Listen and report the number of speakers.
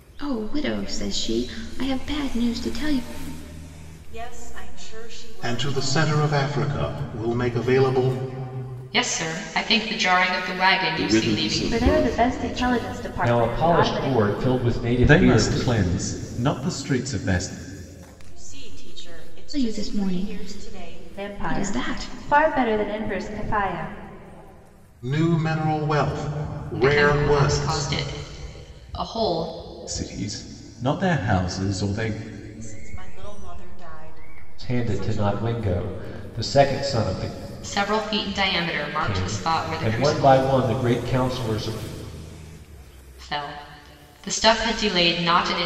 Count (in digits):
8